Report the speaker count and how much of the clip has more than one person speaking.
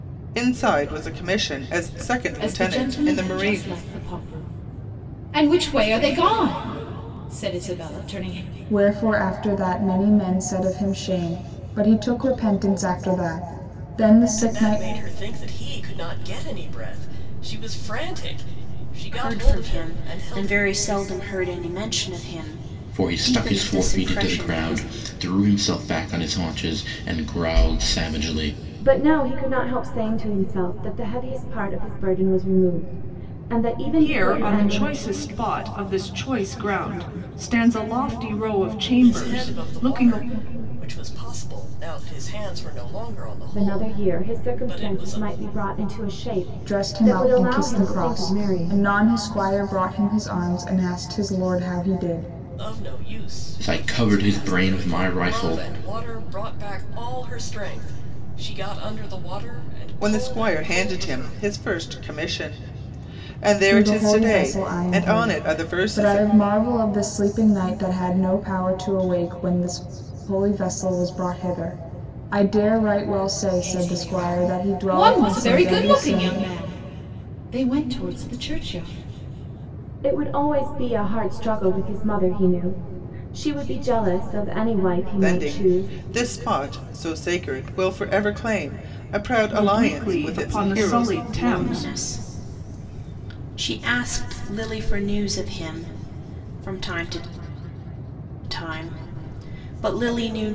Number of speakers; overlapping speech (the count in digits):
8, about 24%